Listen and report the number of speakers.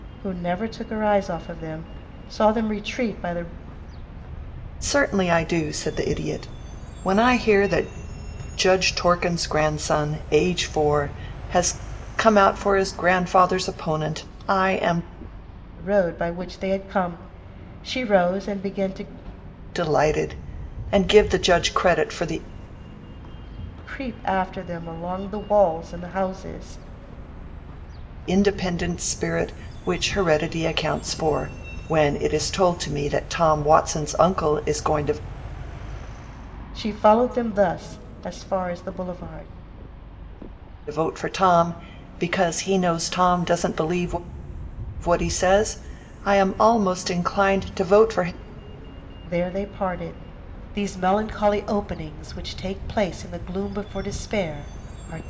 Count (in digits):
2